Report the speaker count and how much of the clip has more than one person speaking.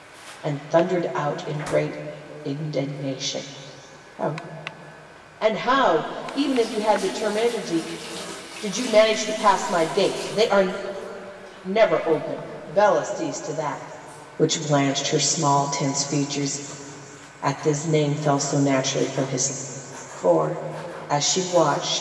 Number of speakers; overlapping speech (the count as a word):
one, no overlap